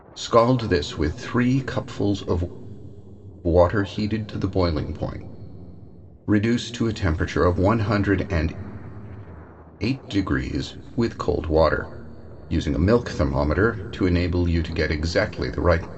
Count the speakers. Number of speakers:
one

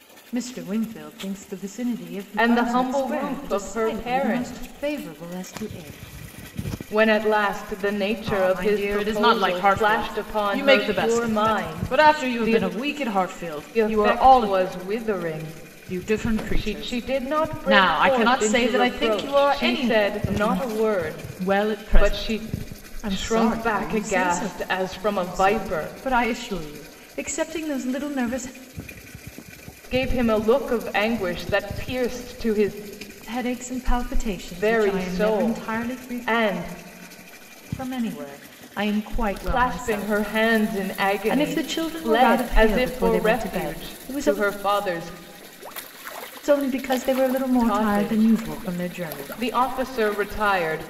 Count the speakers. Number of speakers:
two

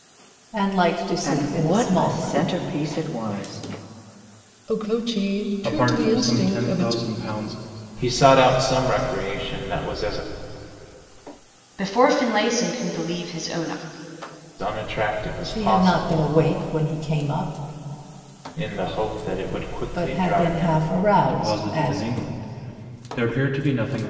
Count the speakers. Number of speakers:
six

